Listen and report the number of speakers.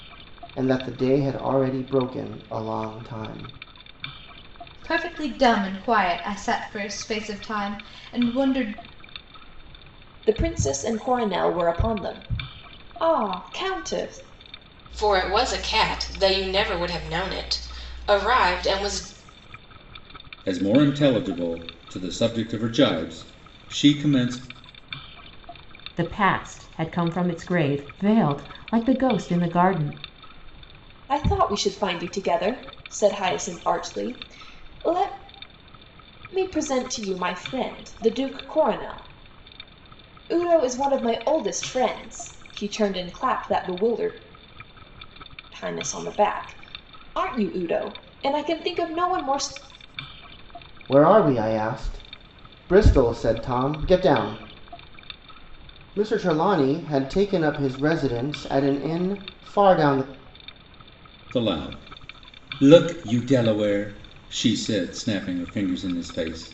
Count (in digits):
6